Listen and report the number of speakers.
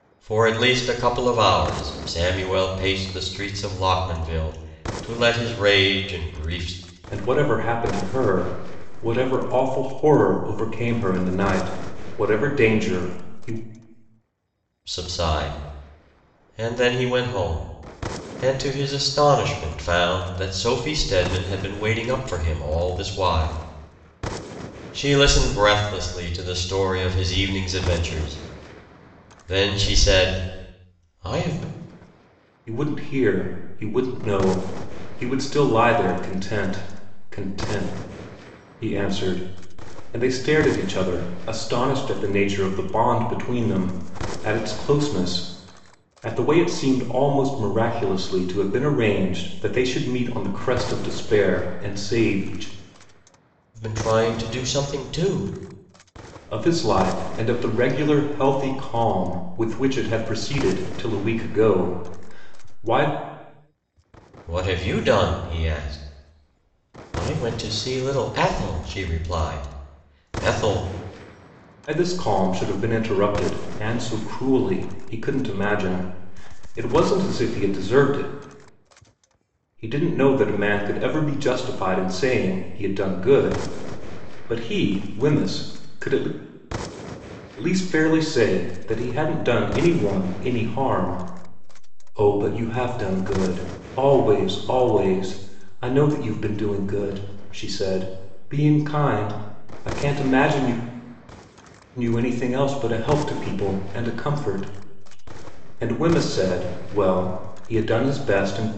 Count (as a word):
two